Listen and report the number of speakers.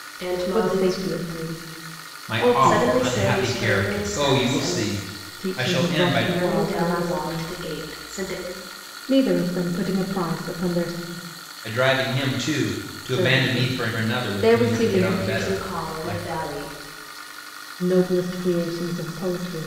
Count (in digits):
3